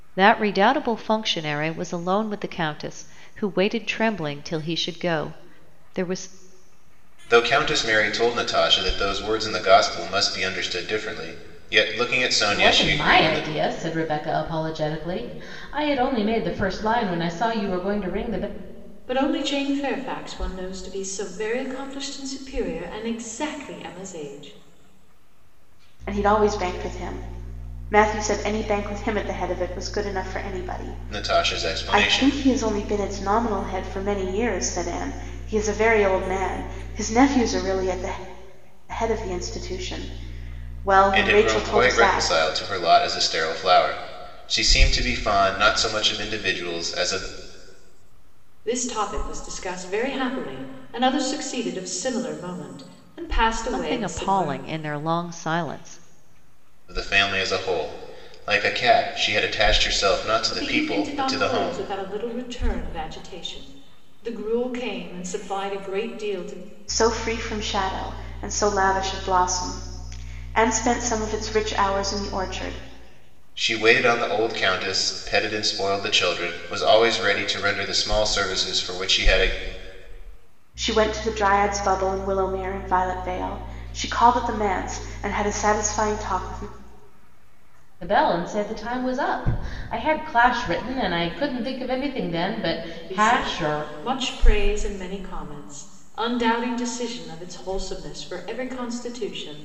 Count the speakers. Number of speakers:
five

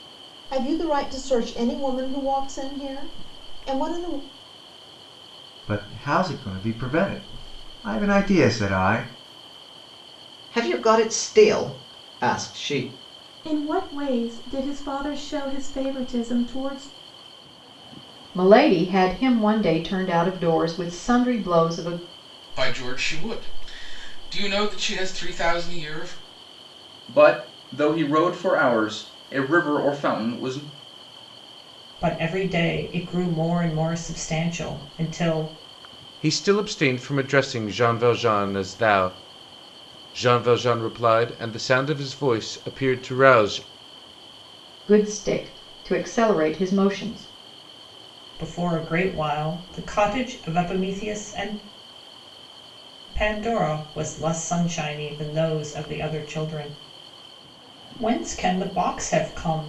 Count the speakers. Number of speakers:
nine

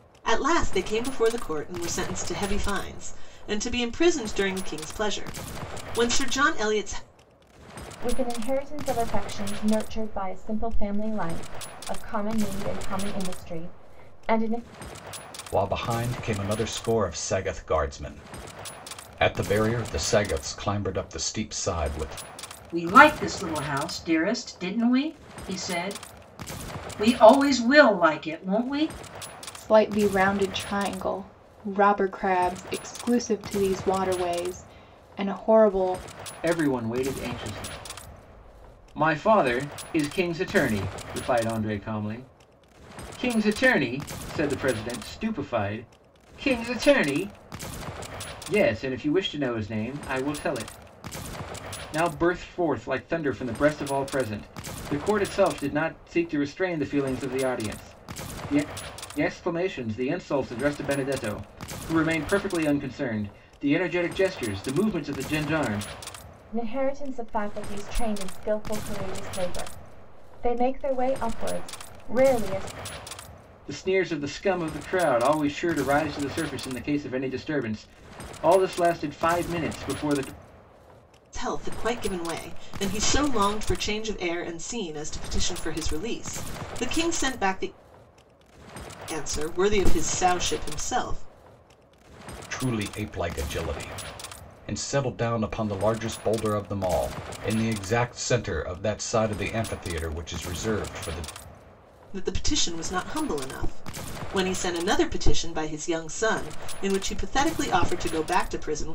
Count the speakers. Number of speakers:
six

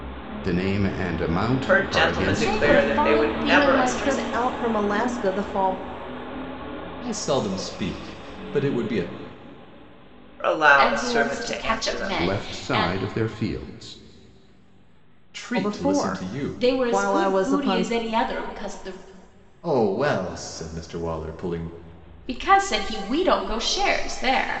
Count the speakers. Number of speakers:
five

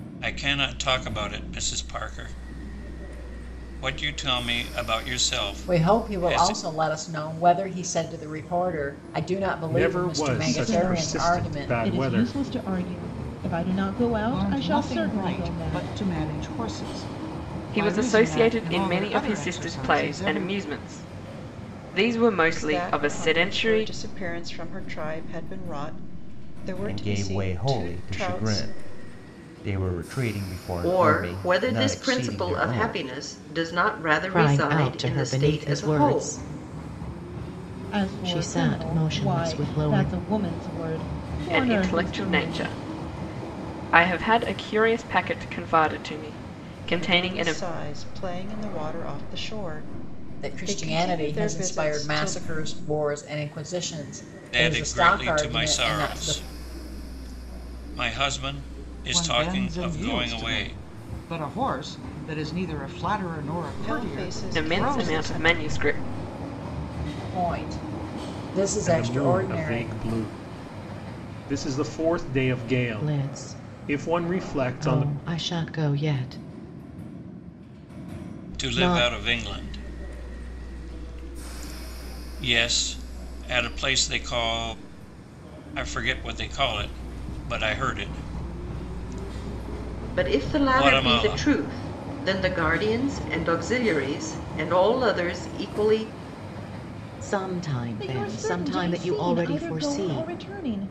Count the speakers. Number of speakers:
ten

